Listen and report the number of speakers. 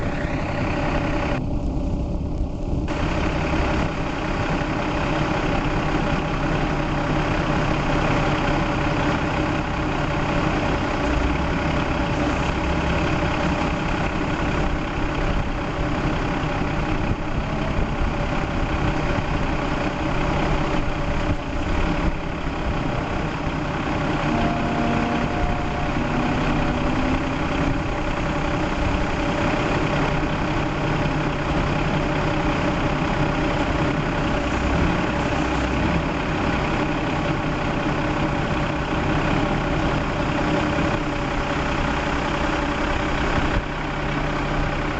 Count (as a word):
zero